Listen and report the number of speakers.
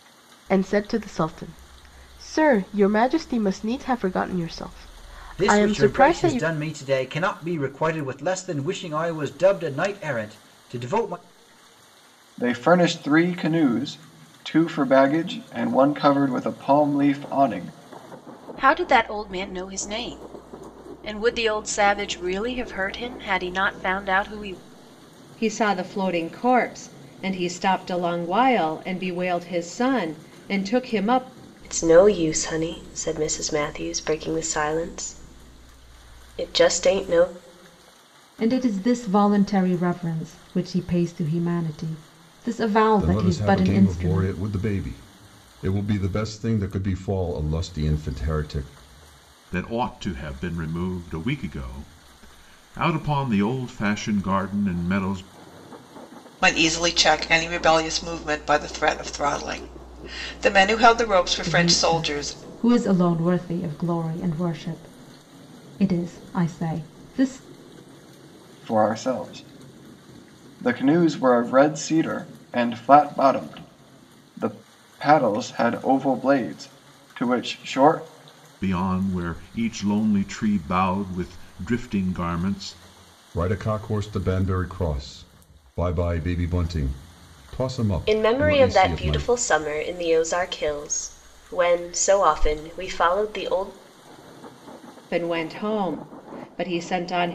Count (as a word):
ten